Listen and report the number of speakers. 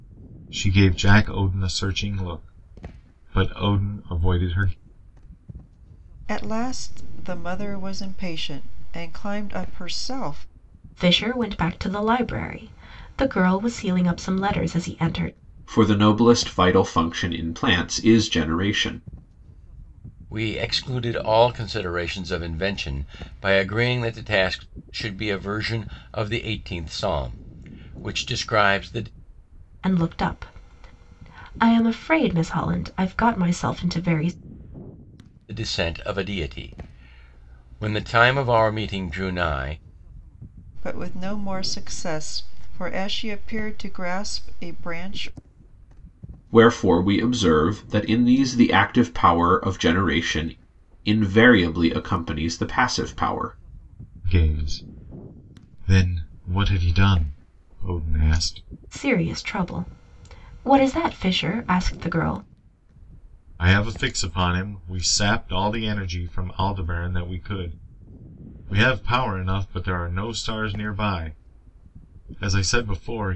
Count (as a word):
five